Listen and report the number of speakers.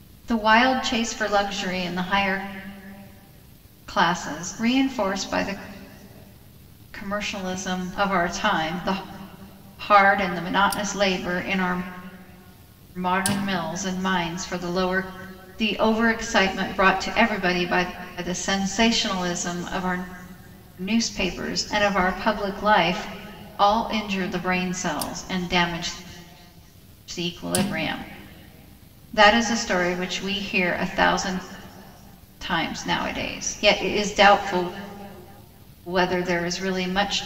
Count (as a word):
one